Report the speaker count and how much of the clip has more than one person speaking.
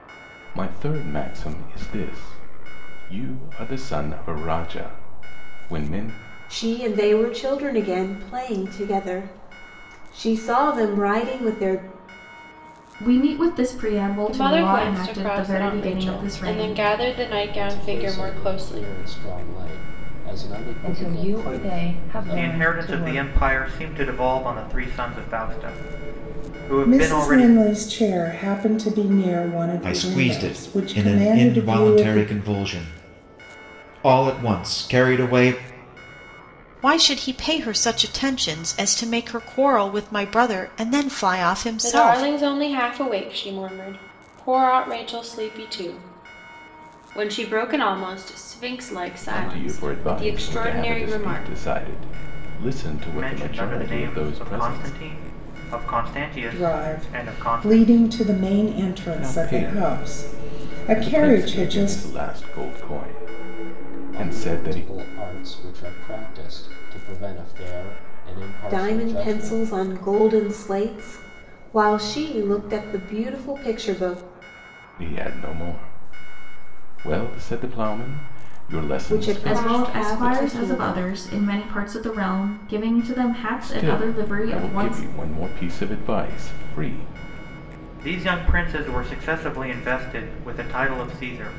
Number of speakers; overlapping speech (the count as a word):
ten, about 27%